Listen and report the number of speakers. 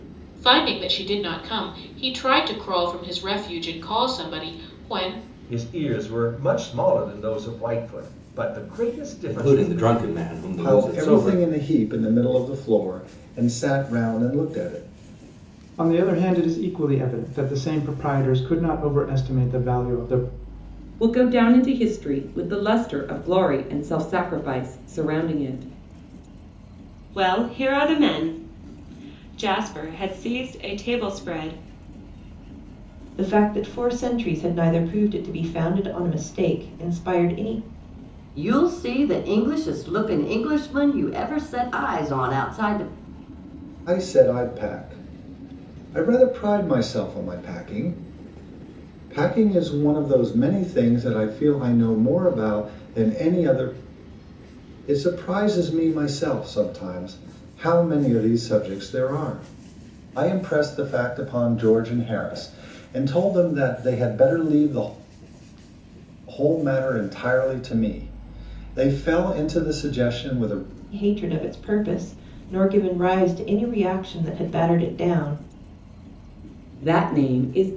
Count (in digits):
9